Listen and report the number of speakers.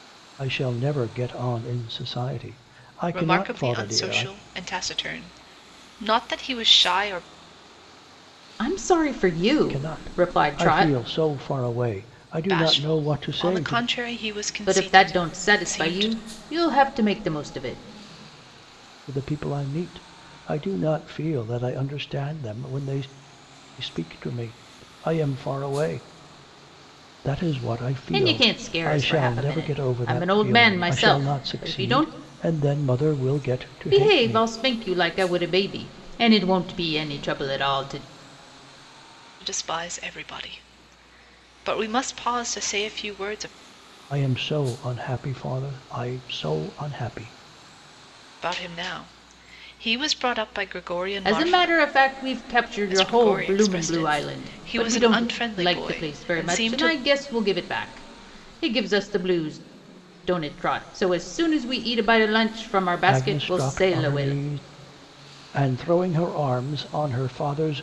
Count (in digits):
3